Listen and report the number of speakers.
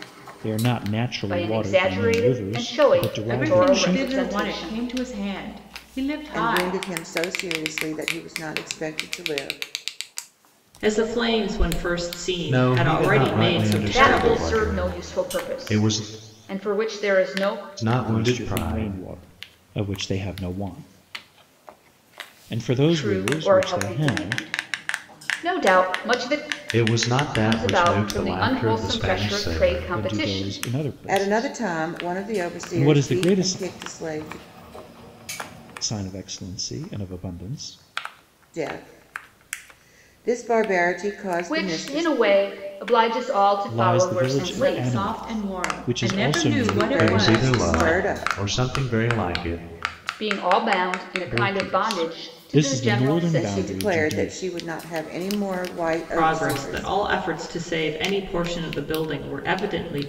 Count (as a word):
six